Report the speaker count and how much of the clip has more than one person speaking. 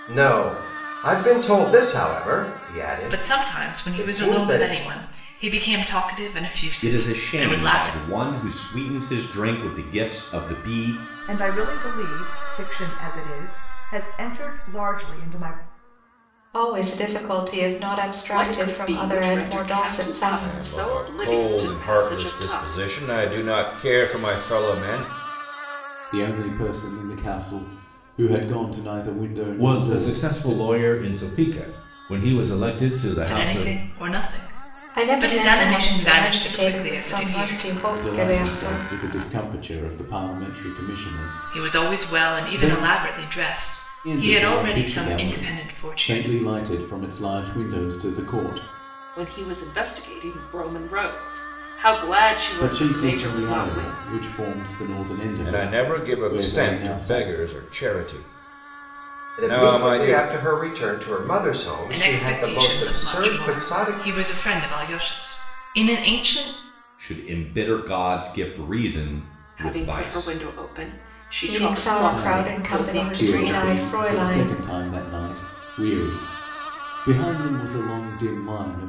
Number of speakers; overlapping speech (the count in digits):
9, about 34%